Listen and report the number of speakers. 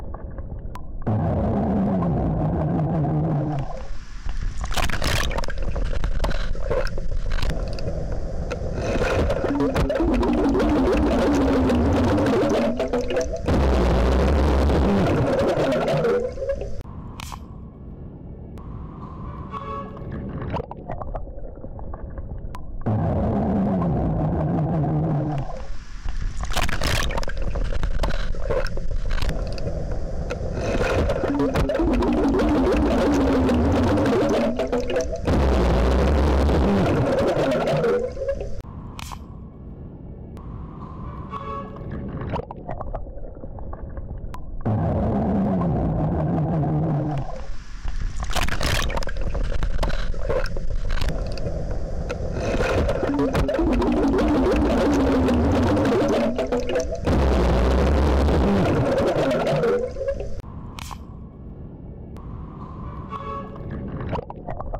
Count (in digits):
0